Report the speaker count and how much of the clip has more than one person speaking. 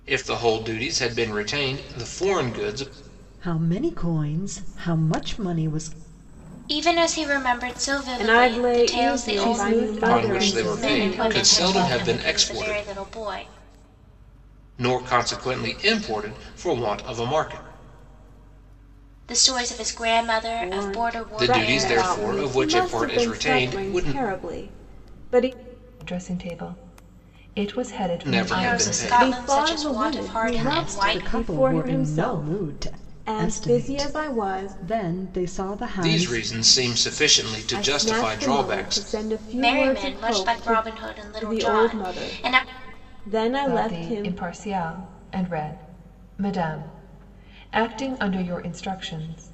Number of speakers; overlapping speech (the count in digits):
5, about 39%